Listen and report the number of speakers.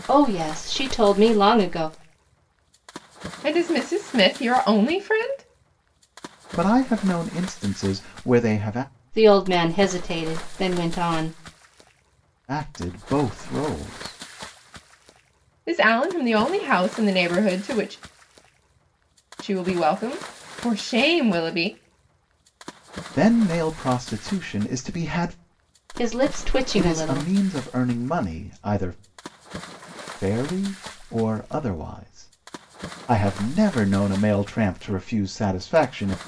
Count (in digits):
3